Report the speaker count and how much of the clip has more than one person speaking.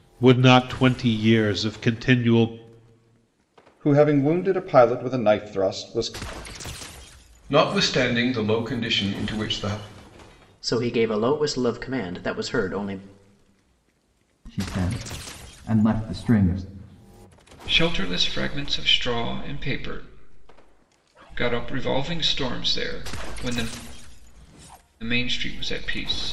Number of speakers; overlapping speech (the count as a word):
six, no overlap